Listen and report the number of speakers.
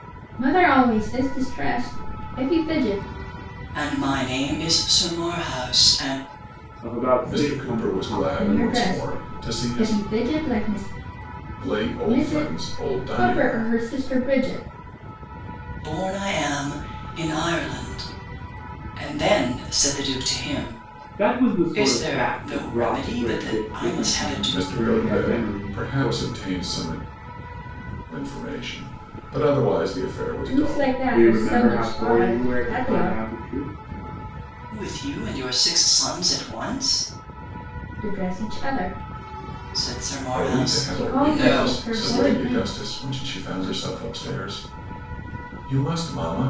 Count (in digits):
4